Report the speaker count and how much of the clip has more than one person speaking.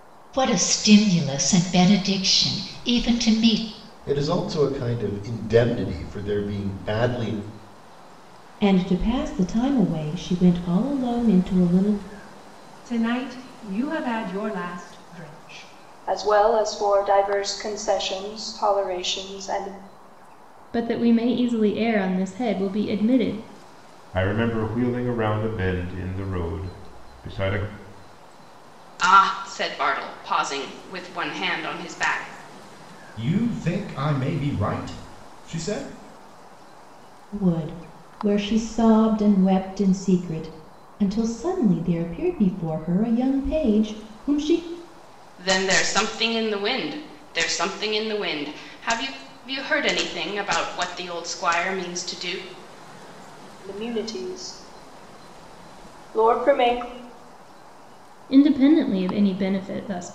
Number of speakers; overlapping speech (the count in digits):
9, no overlap